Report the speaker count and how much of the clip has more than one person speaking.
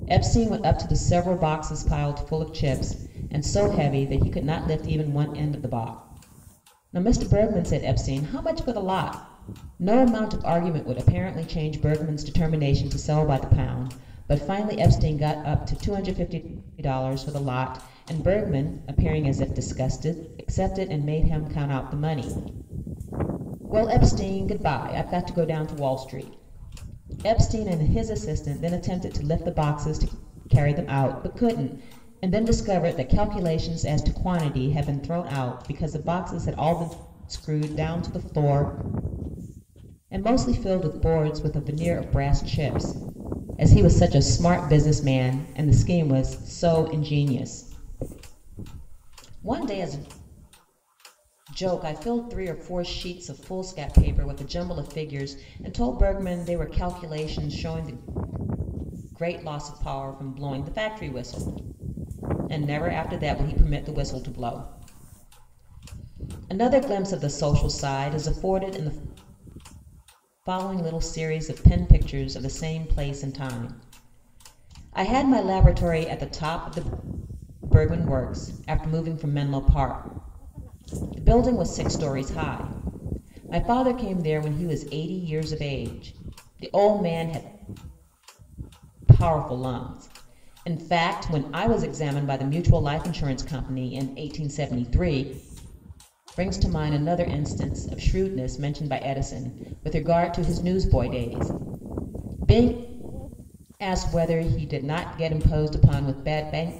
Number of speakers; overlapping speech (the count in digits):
1, no overlap